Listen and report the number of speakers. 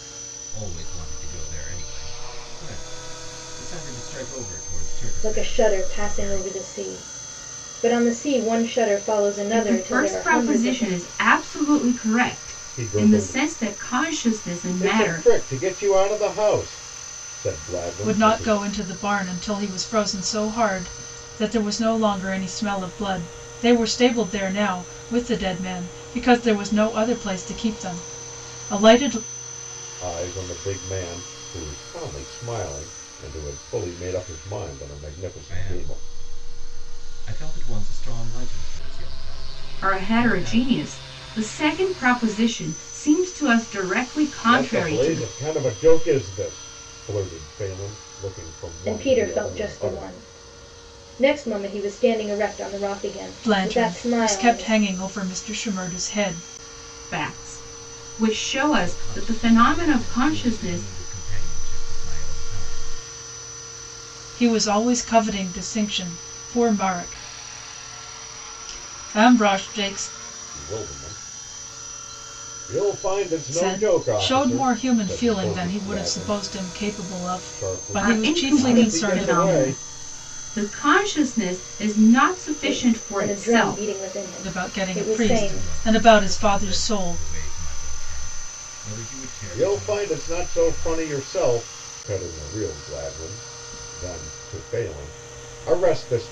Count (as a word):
five